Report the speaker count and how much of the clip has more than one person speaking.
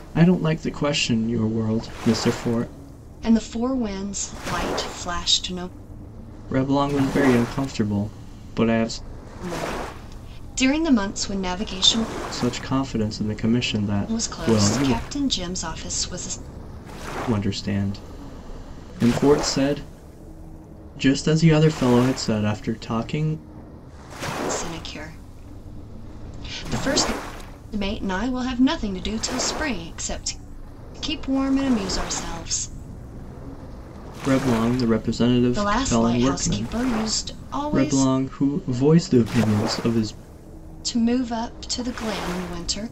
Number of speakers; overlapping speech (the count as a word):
two, about 6%